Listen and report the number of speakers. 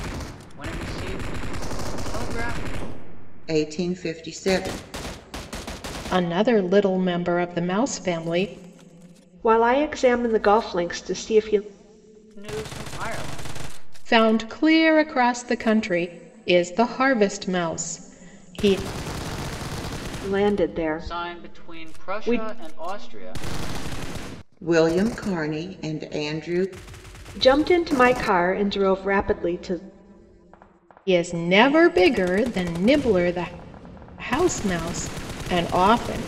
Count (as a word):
four